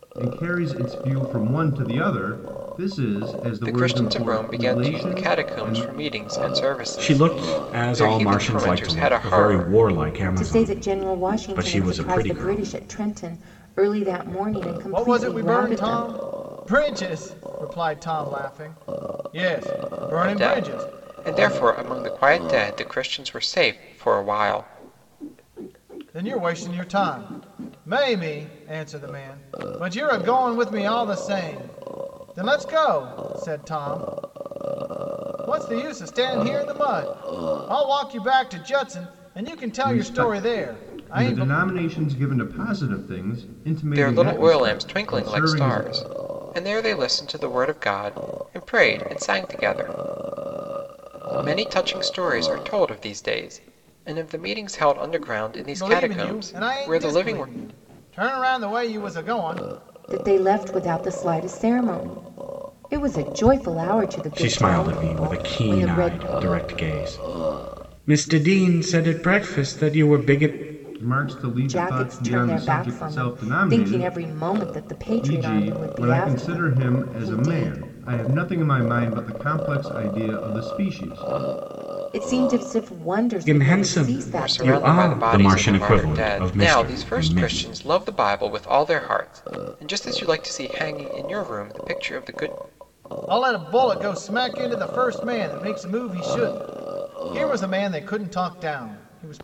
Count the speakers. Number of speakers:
5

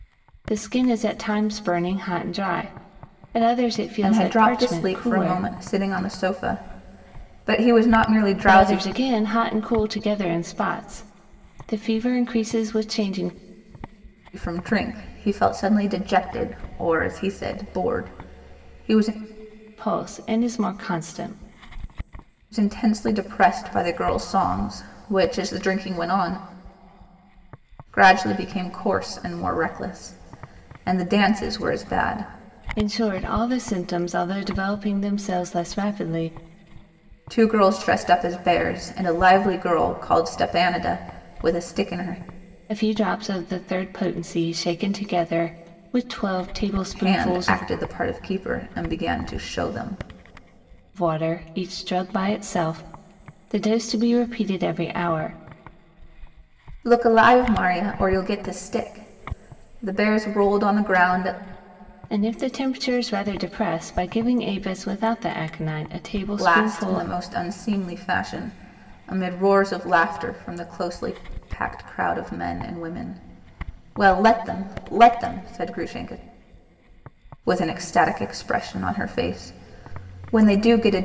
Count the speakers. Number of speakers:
2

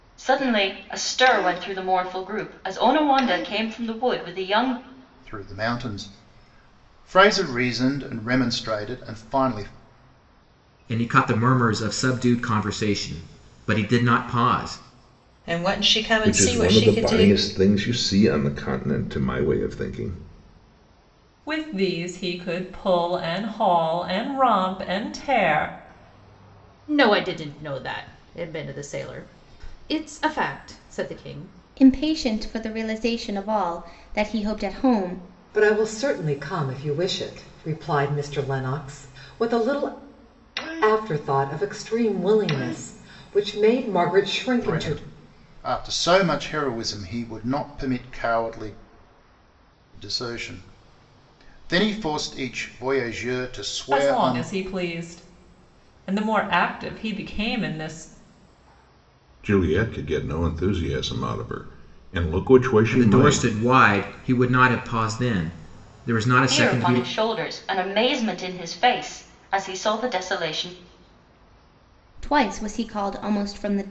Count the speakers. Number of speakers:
9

